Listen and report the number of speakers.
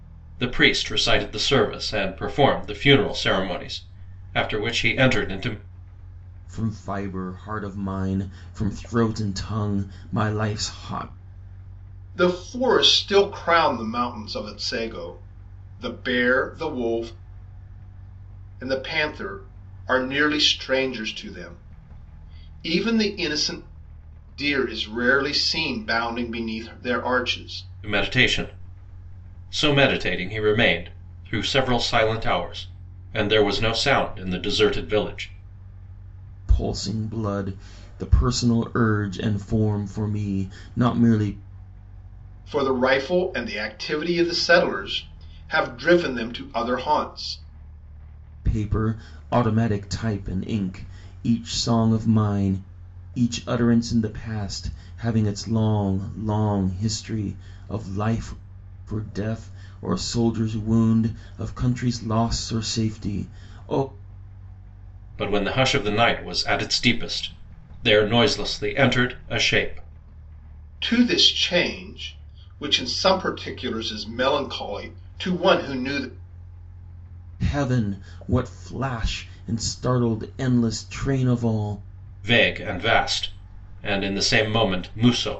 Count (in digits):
3